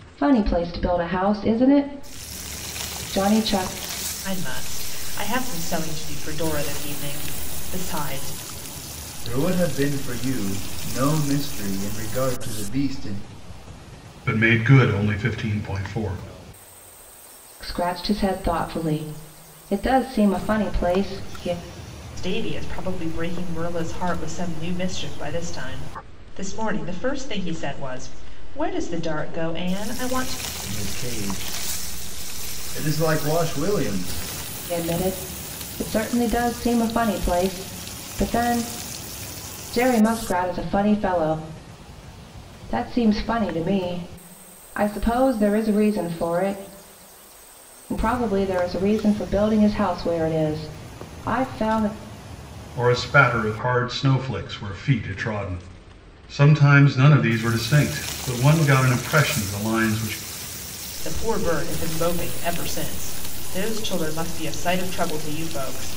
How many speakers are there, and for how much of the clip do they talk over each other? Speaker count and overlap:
four, no overlap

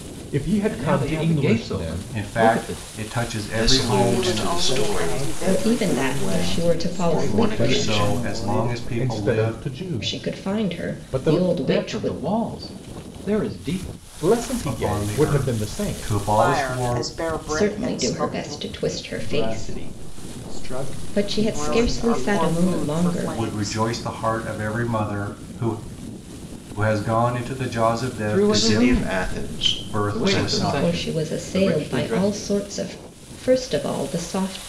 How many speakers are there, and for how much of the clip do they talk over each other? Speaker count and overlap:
seven, about 59%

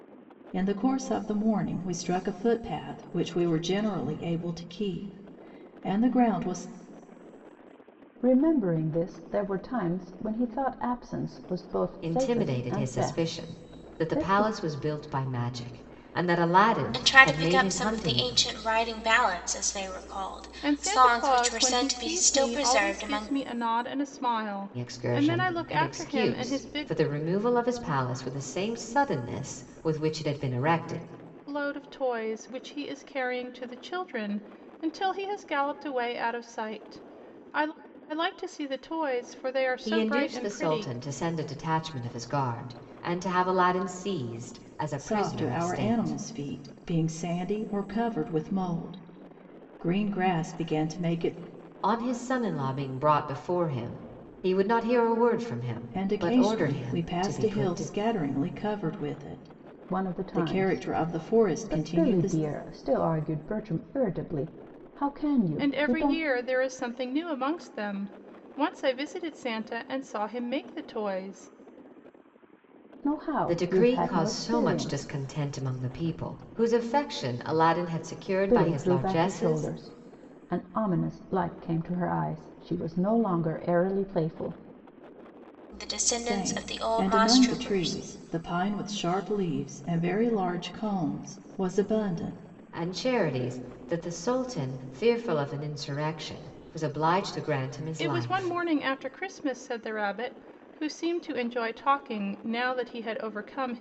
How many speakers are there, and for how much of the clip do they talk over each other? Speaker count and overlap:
five, about 21%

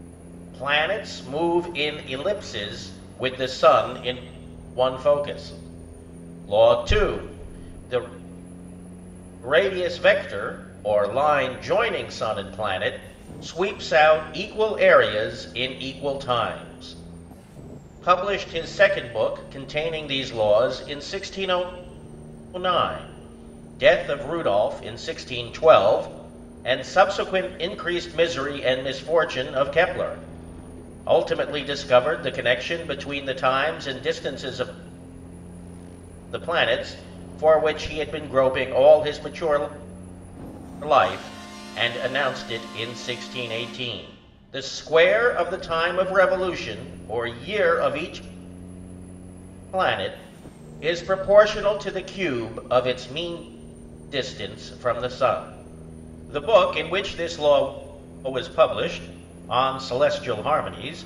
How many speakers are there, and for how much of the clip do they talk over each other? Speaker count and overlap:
one, no overlap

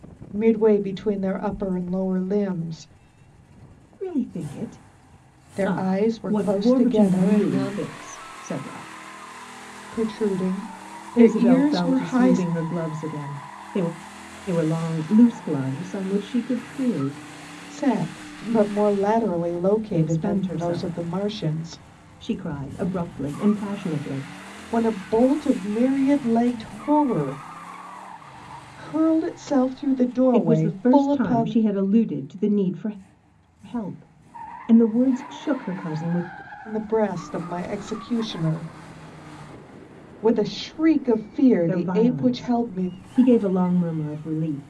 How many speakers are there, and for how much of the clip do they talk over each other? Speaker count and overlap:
two, about 16%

